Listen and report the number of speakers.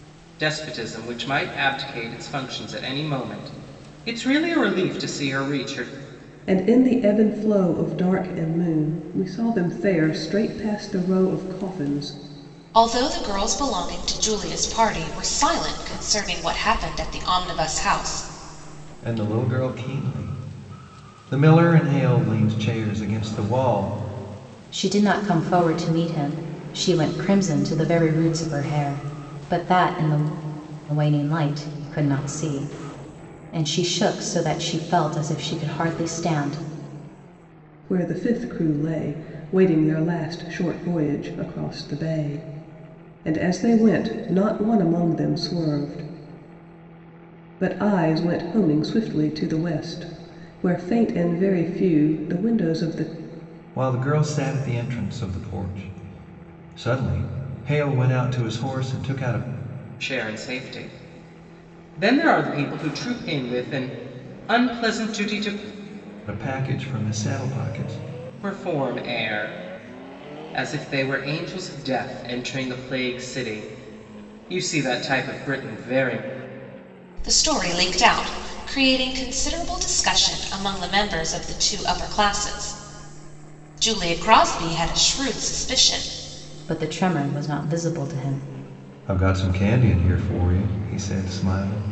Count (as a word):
five